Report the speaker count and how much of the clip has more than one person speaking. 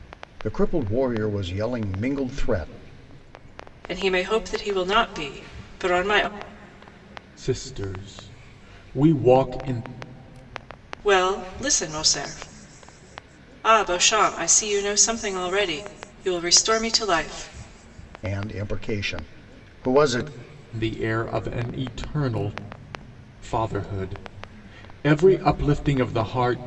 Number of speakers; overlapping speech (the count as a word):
three, no overlap